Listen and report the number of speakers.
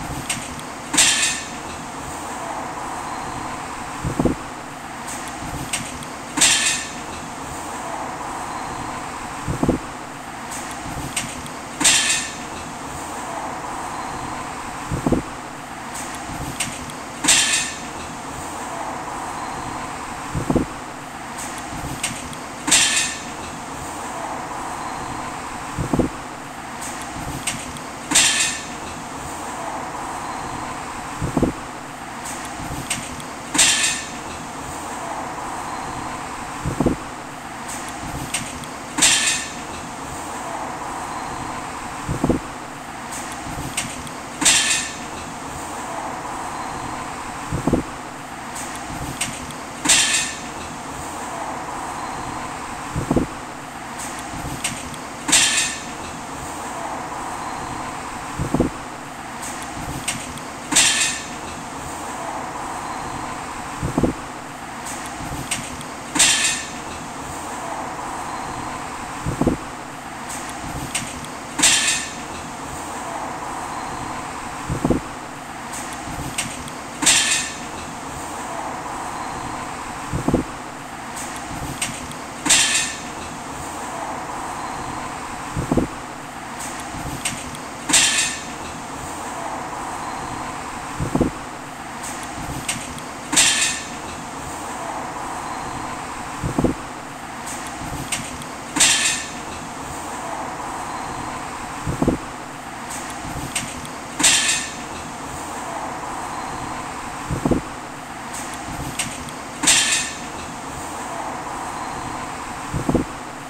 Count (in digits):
0